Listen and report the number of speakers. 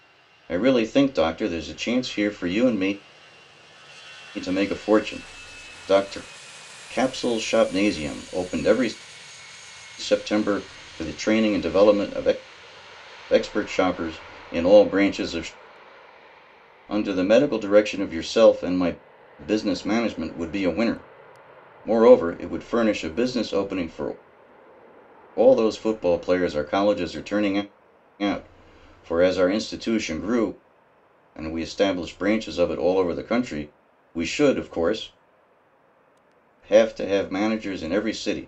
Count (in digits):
1